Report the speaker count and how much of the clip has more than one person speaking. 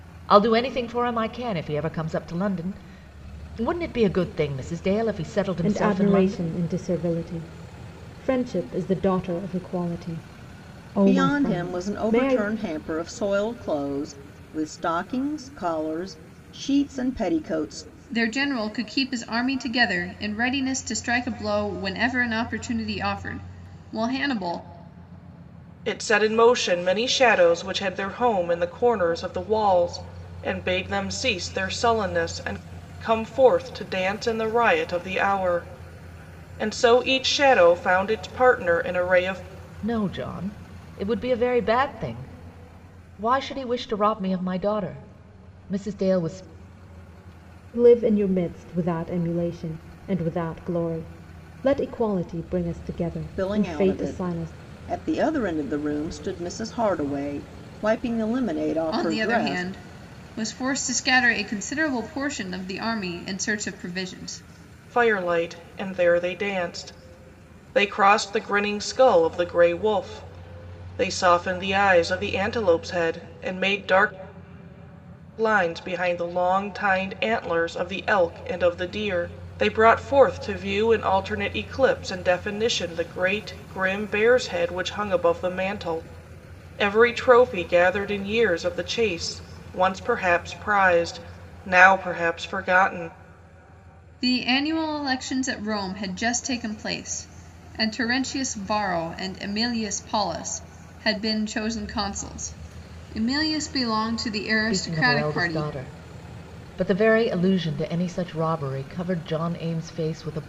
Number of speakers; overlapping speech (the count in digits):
5, about 5%